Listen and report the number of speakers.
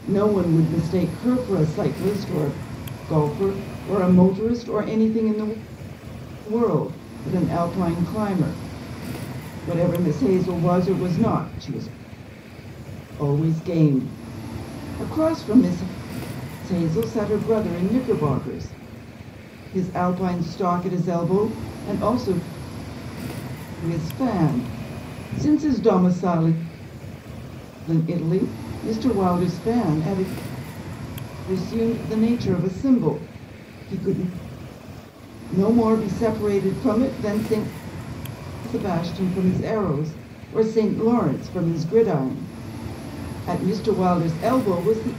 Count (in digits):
1